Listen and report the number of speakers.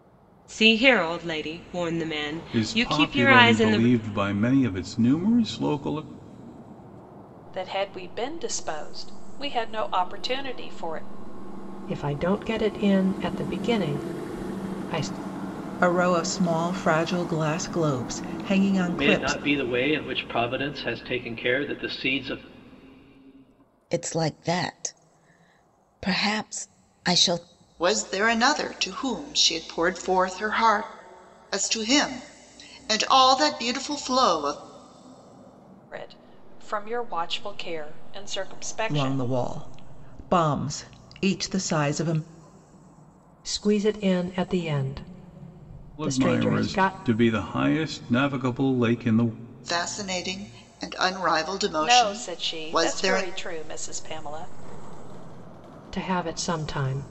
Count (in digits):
8